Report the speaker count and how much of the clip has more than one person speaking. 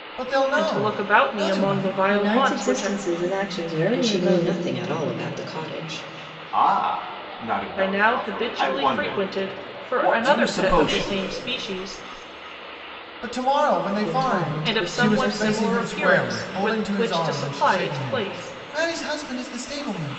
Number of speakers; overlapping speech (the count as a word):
five, about 54%